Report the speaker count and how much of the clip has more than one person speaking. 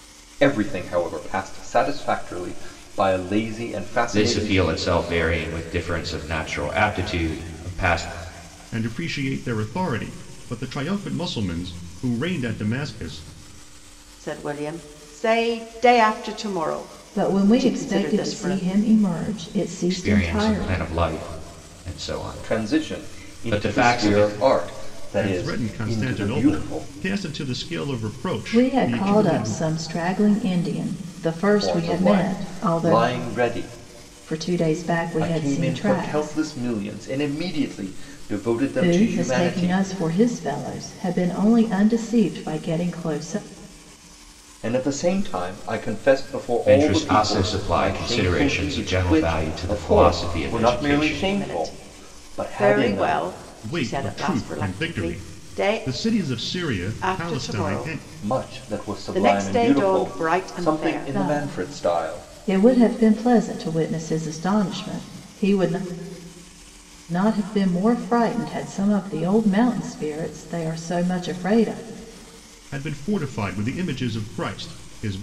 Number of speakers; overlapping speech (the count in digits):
5, about 34%